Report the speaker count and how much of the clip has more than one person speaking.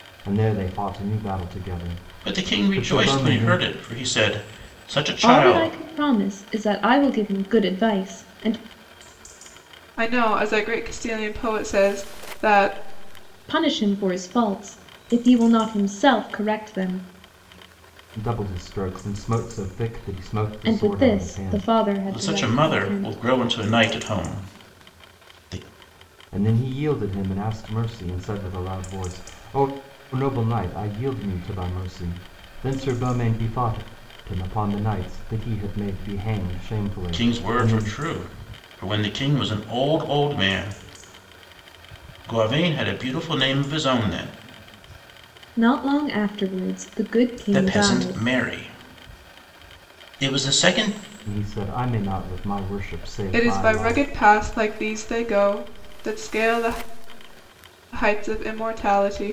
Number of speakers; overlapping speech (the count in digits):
4, about 12%